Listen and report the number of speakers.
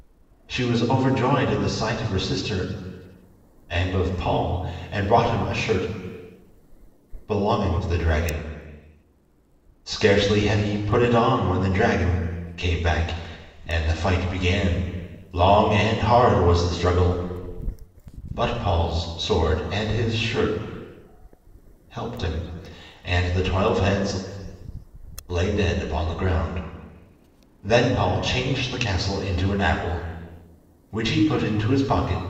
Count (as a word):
one